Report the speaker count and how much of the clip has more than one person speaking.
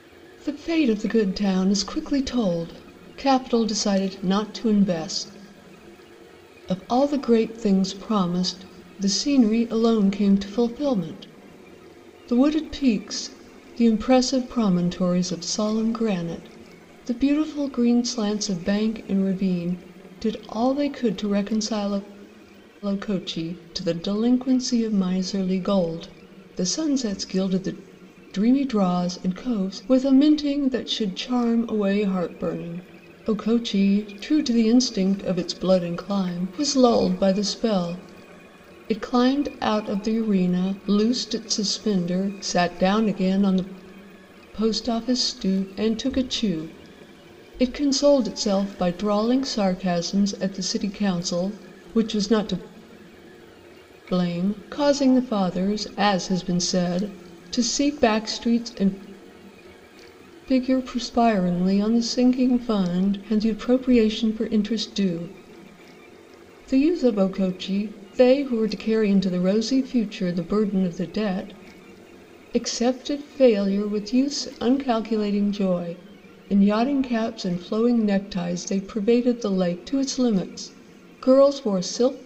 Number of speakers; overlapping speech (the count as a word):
one, no overlap